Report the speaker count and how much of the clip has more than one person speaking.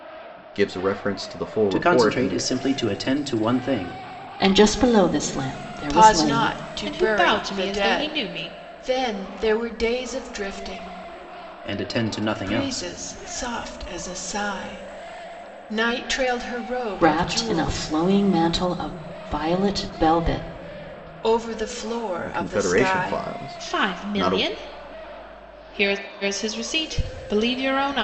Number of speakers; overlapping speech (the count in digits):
5, about 22%